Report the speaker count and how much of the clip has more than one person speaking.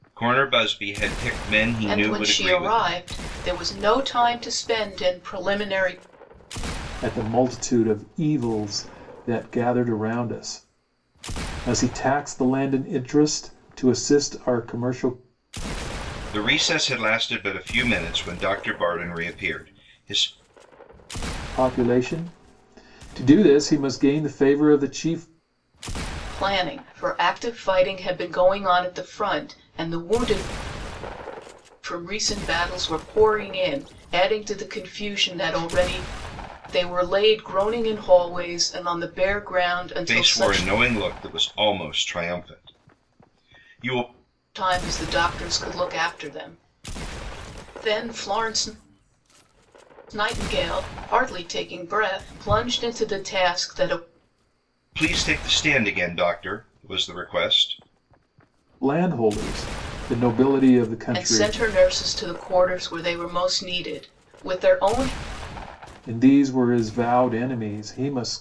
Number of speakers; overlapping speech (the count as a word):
three, about 3%